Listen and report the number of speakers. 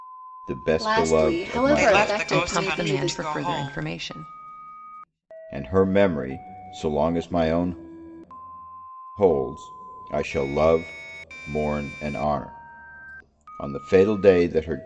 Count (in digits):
4